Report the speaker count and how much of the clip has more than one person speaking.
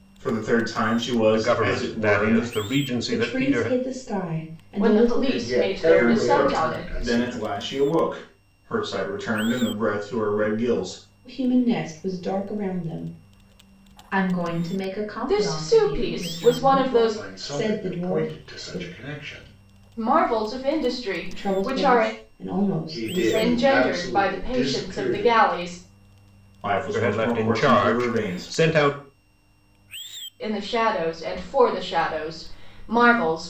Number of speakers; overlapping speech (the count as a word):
five, about 40%